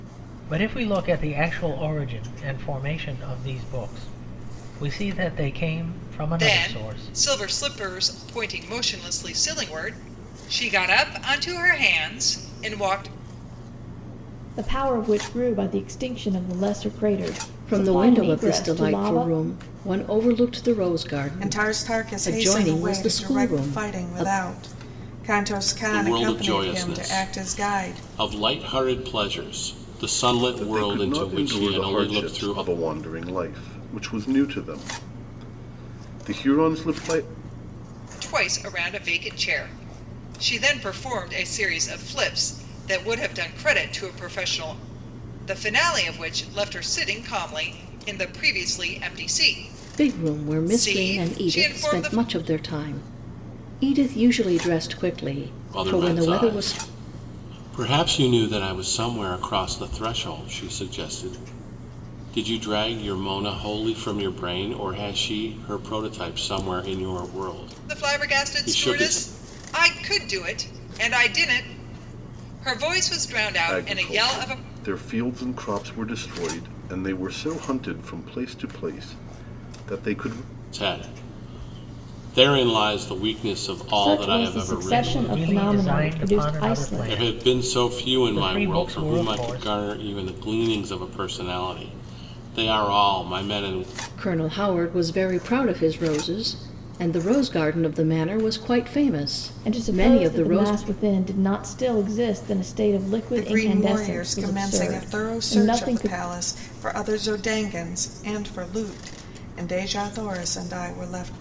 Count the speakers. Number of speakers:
seven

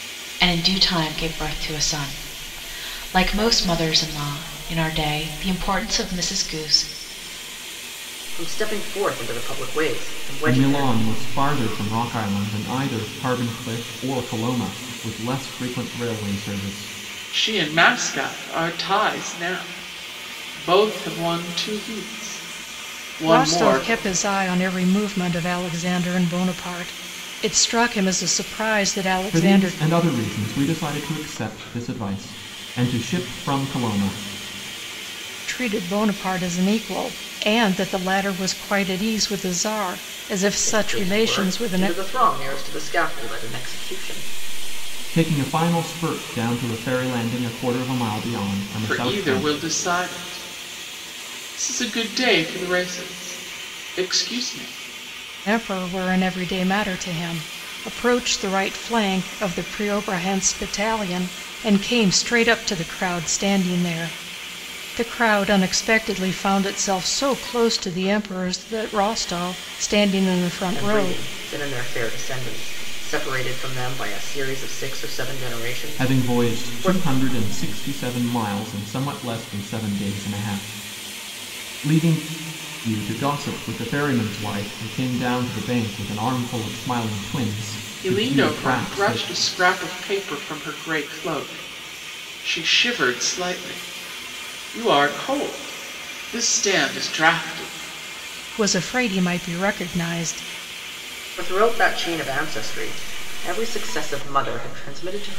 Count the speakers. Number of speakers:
five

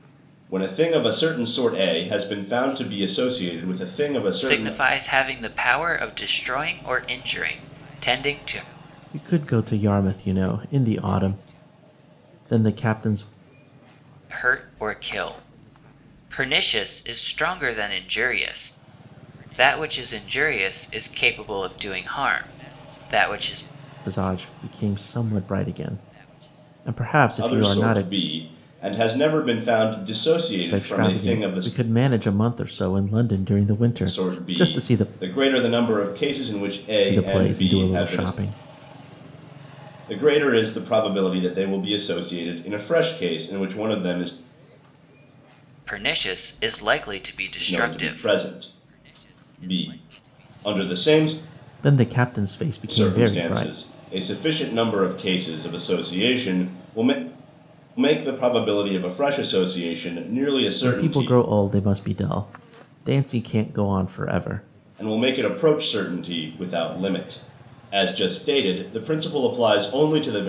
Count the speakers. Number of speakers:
three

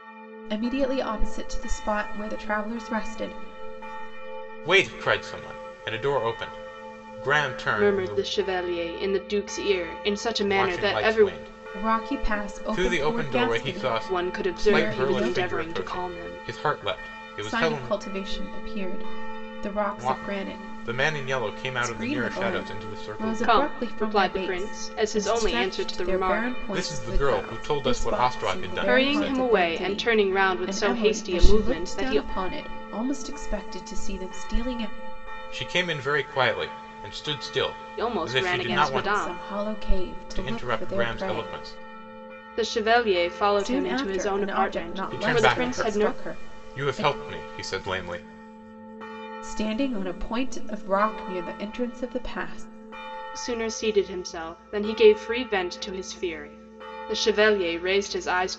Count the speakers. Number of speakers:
three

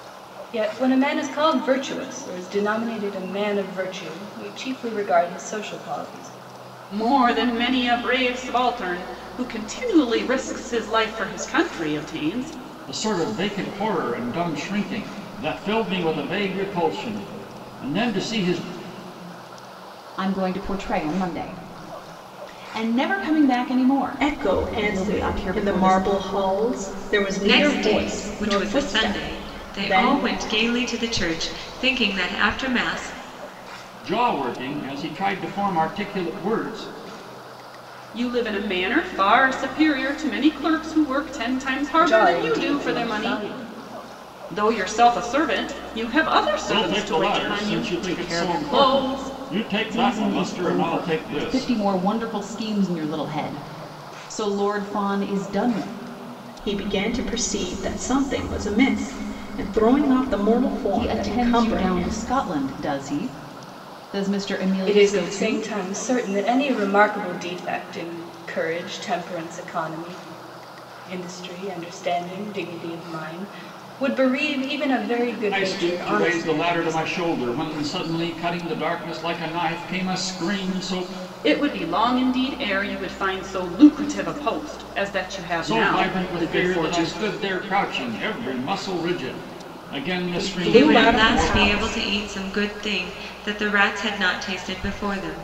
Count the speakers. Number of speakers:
six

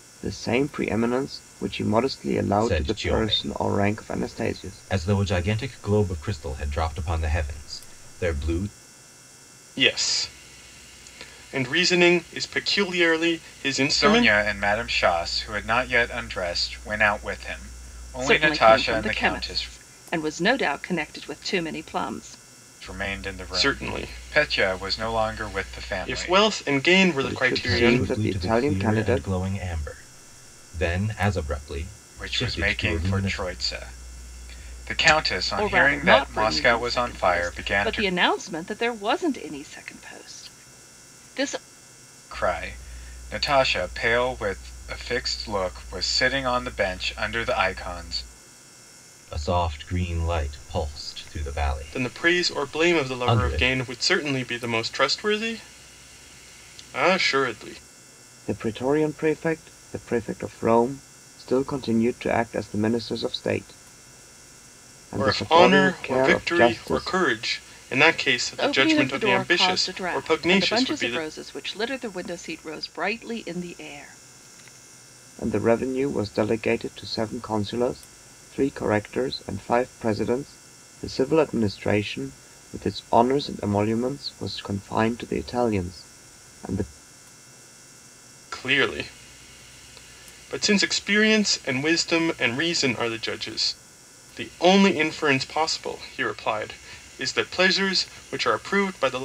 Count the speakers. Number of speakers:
five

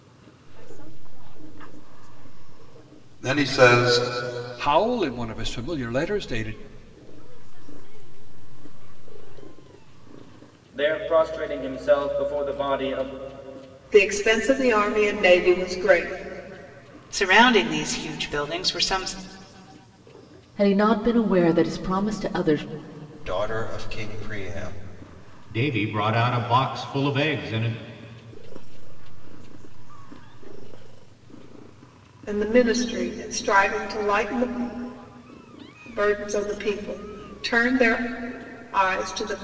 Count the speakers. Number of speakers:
ten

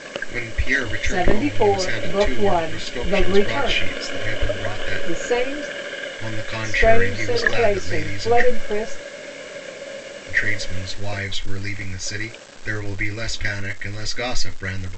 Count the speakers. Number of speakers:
two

